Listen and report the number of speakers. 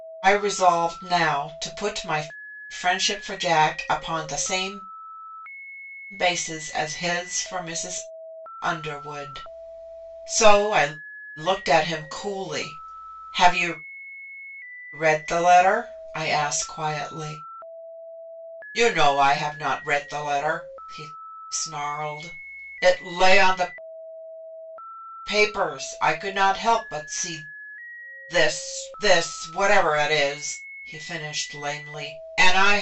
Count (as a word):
one